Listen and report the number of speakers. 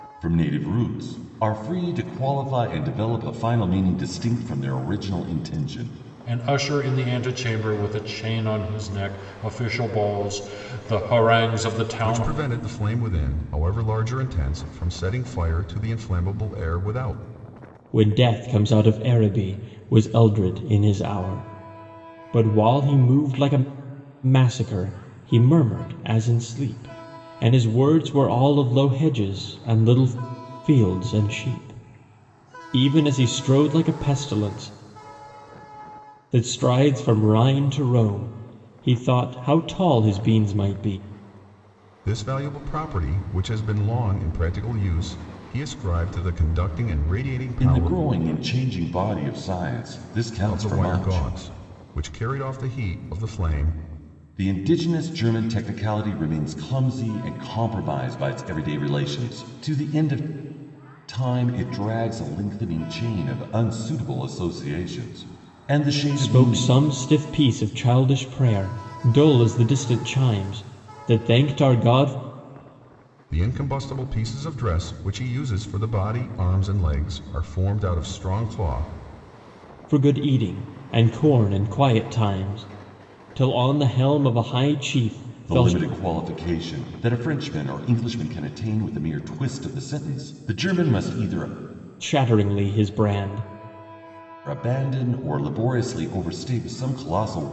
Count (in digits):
4